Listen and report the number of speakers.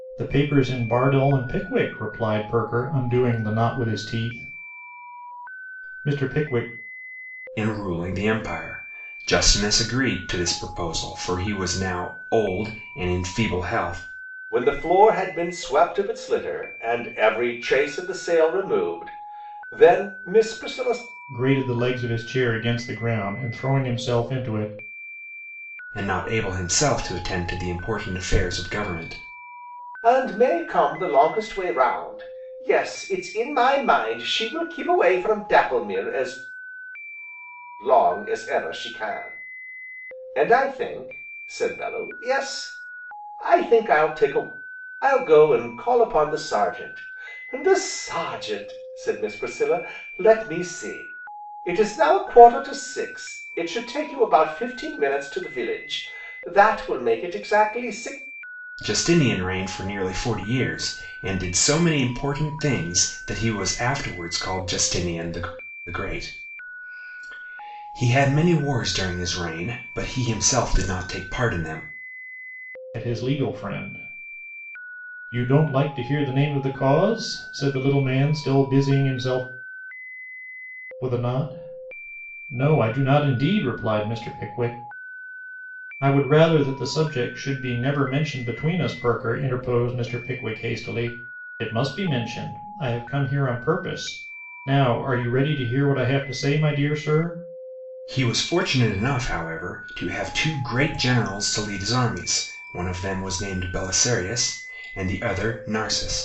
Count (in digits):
3